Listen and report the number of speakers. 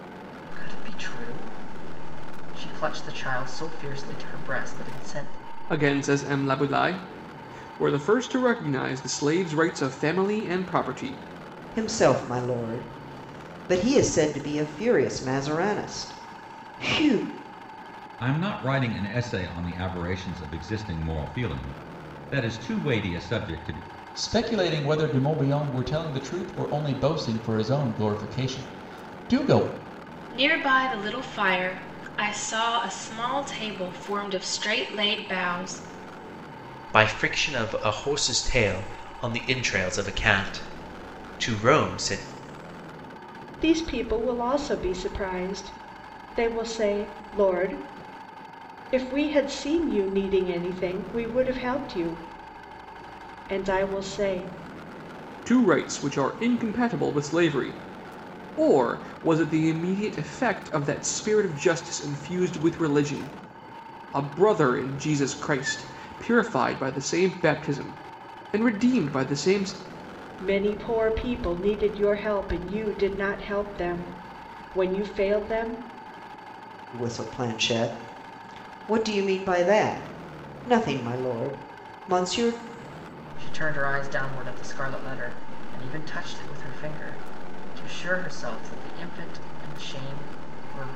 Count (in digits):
8